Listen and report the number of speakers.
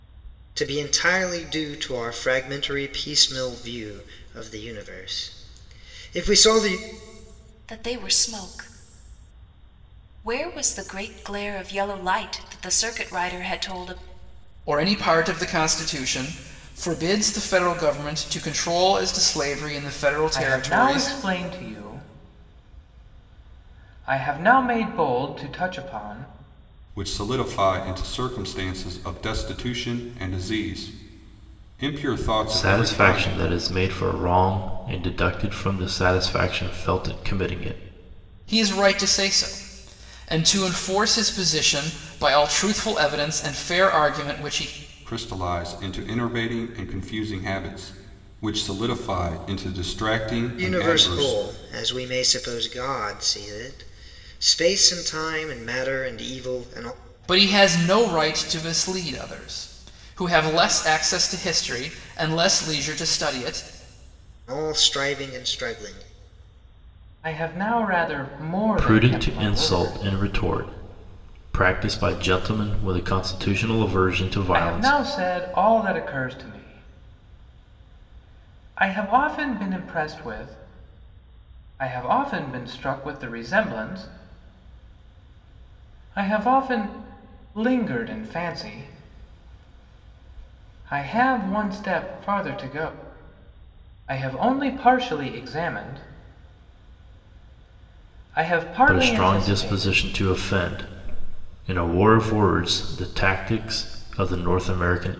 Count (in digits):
6